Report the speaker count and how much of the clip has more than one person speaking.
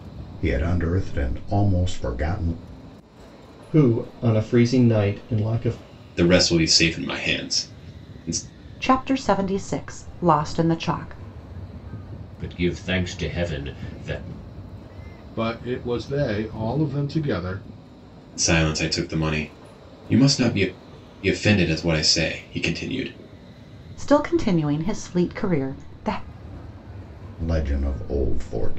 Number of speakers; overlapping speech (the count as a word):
six, no overlap